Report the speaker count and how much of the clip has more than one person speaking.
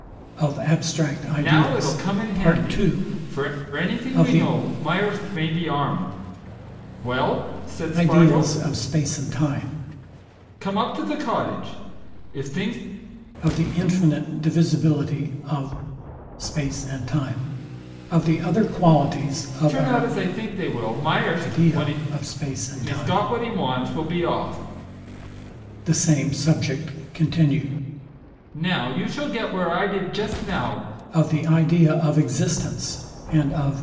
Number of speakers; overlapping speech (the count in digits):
2, about 14%